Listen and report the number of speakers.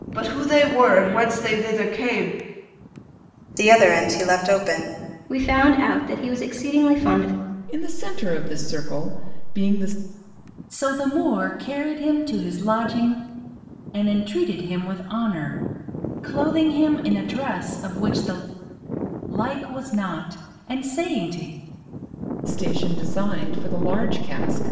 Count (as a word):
five